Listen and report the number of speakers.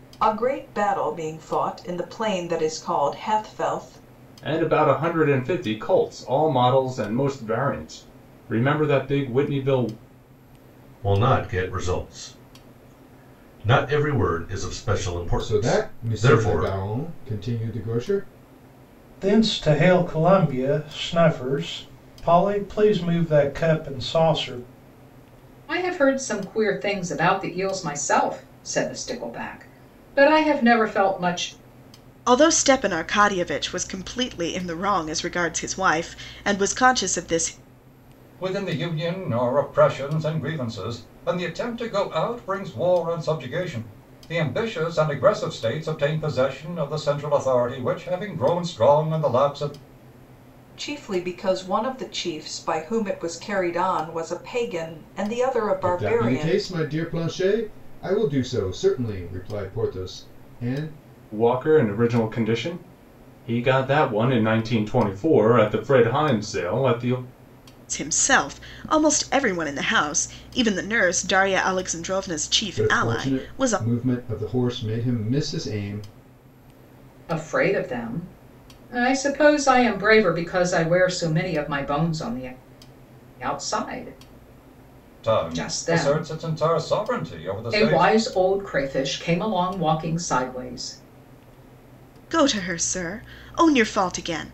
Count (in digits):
8